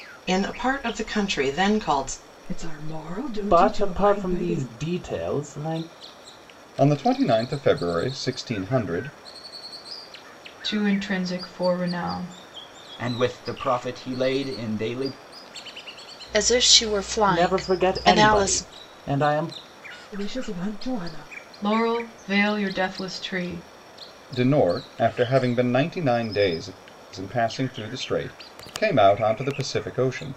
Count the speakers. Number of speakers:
7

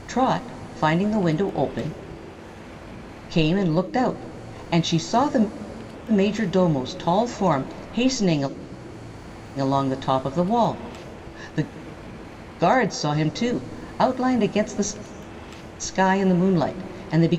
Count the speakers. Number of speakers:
1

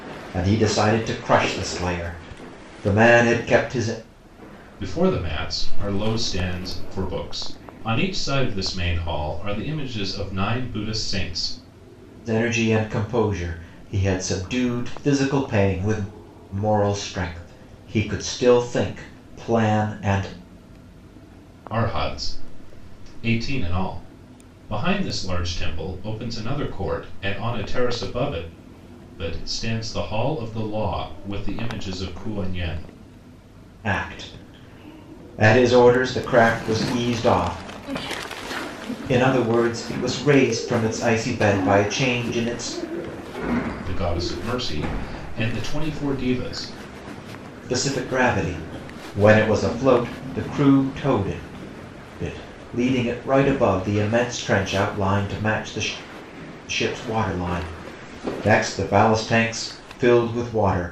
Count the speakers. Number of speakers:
2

